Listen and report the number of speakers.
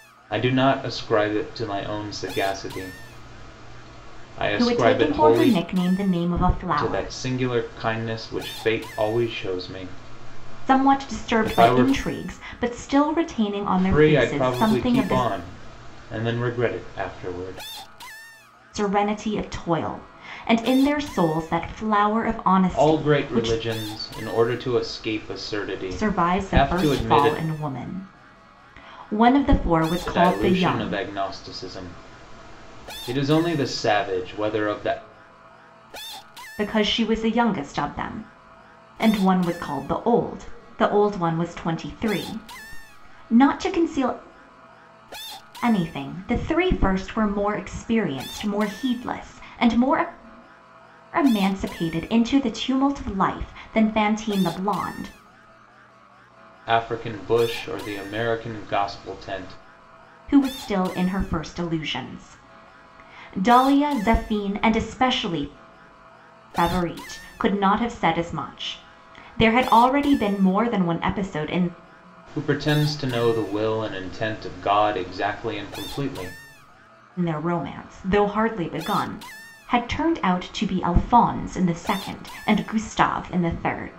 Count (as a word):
two